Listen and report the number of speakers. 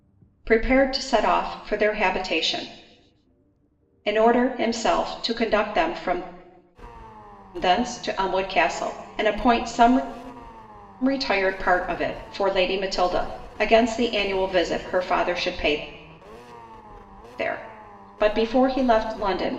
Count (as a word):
one